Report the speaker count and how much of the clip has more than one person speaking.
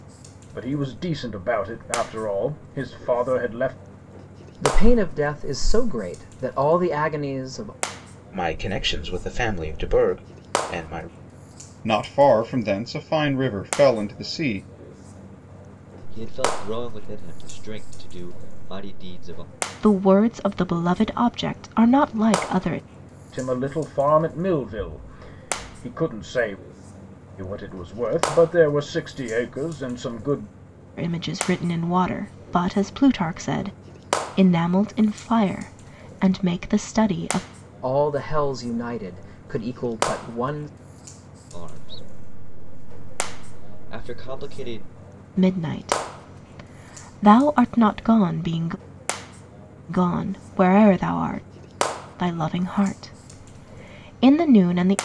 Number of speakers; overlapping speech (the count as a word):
six, no overlap